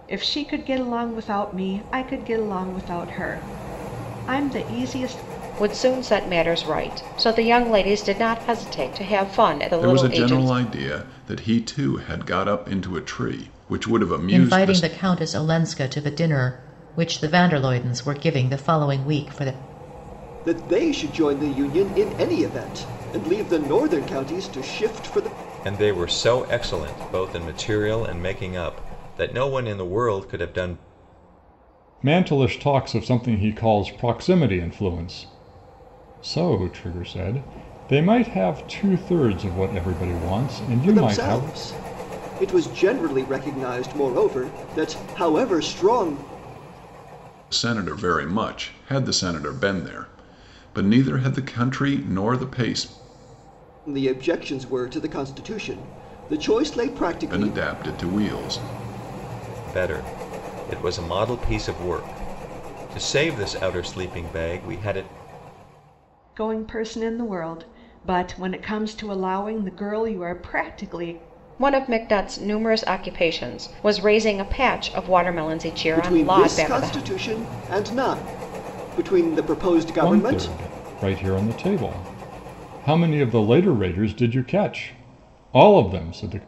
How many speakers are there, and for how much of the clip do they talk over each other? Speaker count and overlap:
seven, about 5%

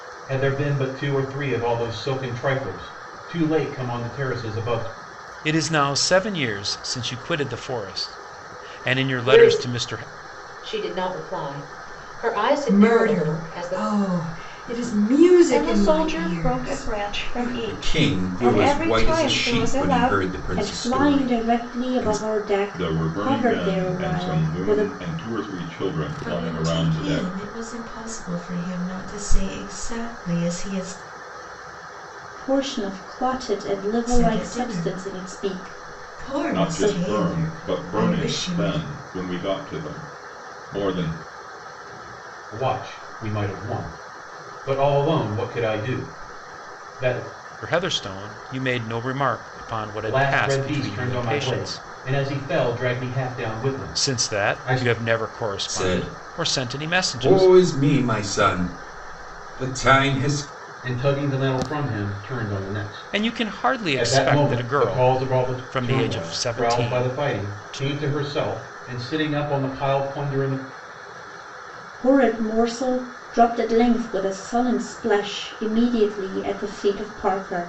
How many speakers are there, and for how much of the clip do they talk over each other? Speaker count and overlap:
nine, about 33%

